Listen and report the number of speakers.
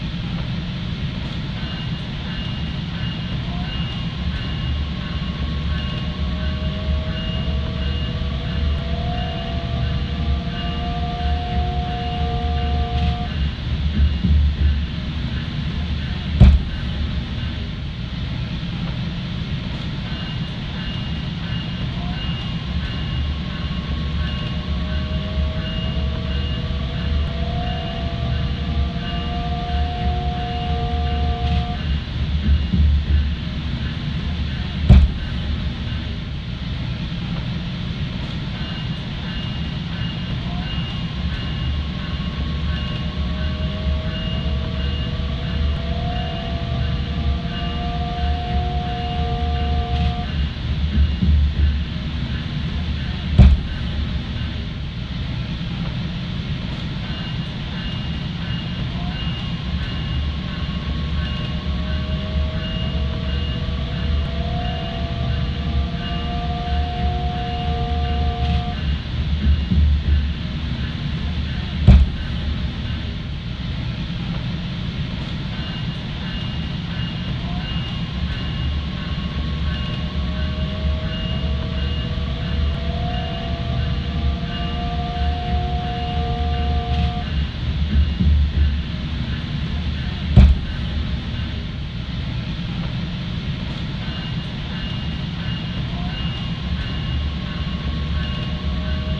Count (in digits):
0